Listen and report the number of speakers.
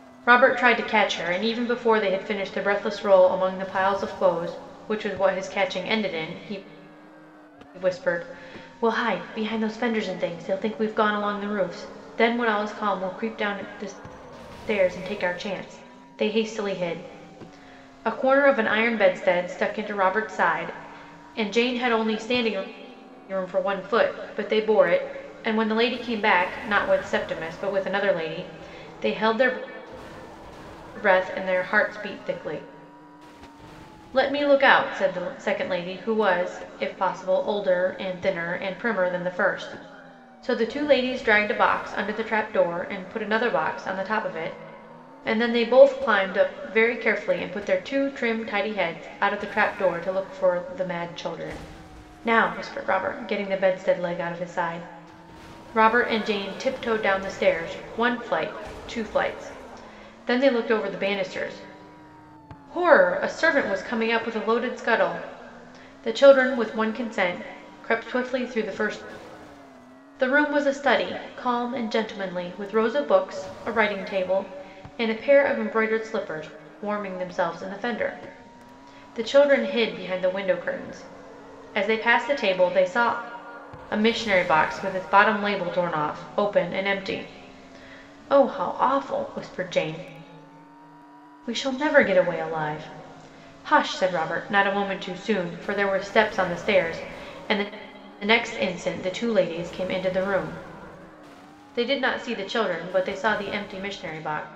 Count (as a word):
one